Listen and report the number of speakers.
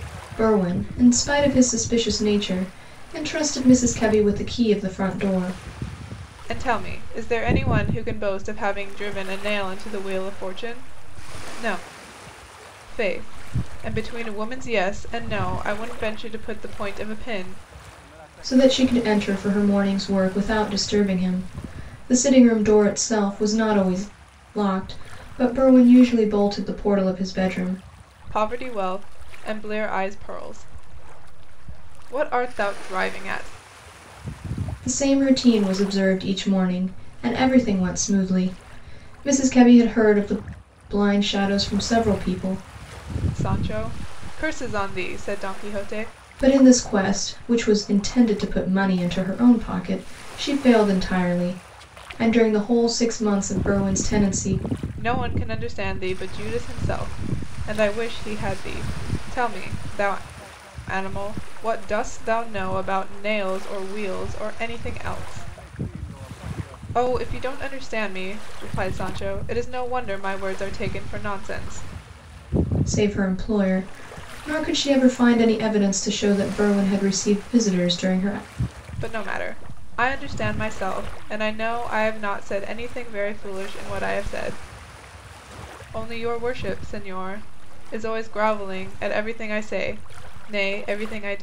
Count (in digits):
2